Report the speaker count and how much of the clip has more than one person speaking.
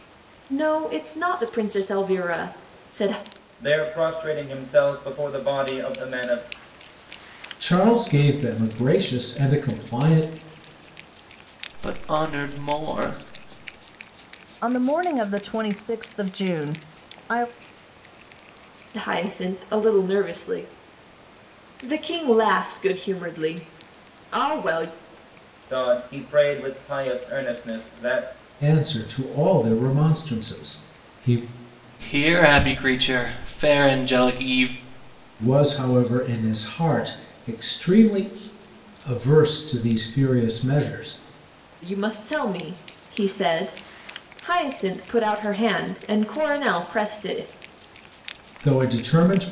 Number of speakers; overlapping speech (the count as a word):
five, no overlap